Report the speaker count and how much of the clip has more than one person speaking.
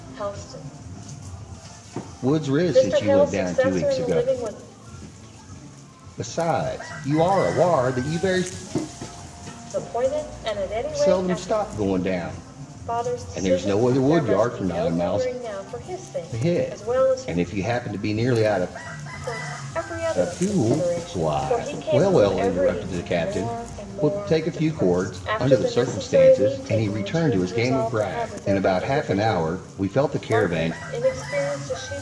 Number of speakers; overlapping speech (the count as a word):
two, about 48%